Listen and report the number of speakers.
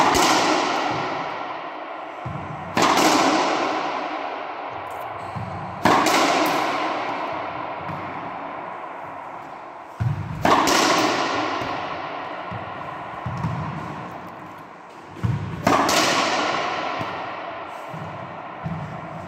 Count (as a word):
zero